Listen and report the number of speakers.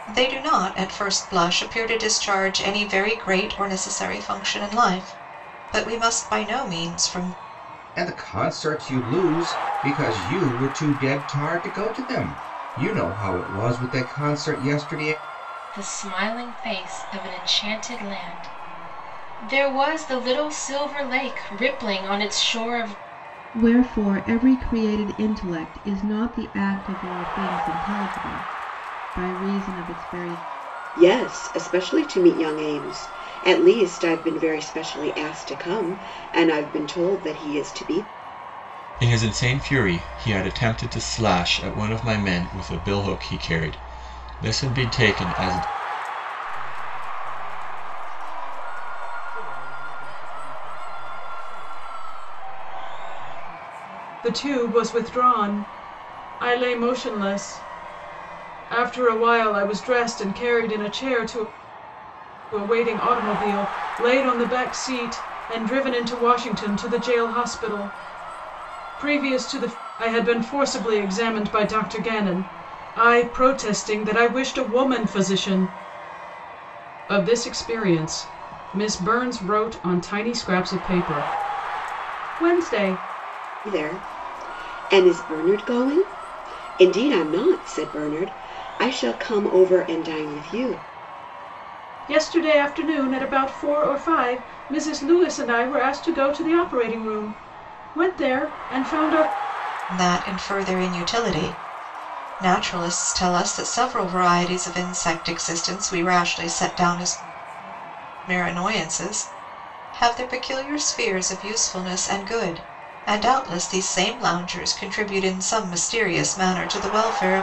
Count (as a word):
eight